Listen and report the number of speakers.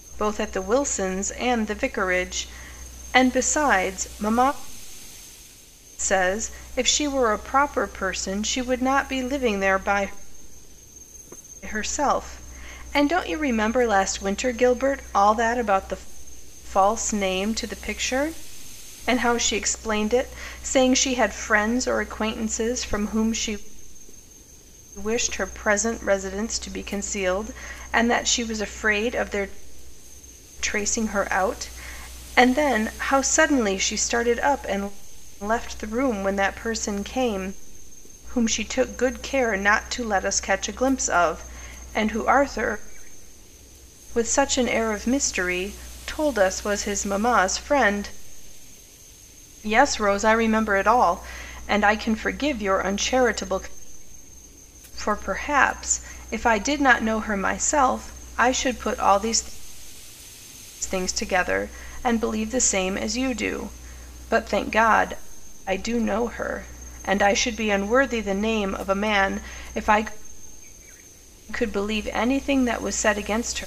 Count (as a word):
one